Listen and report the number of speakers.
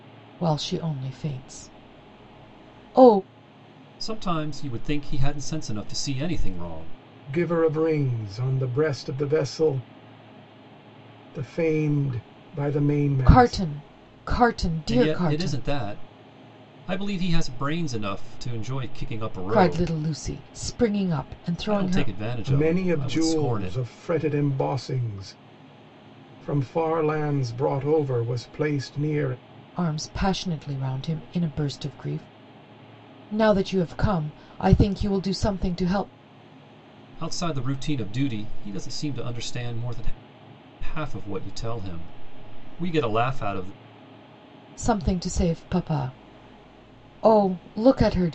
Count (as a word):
three